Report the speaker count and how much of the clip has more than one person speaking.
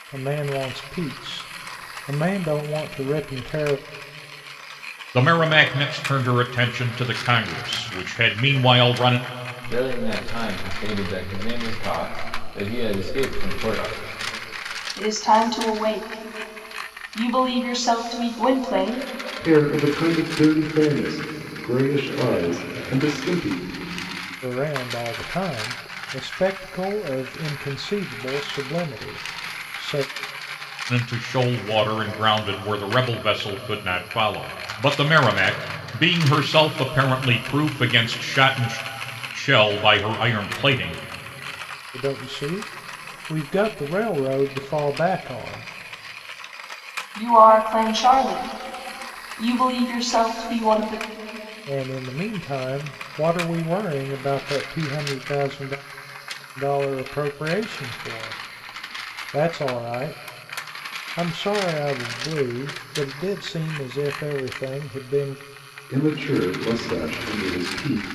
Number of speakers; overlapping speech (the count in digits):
5, no overlap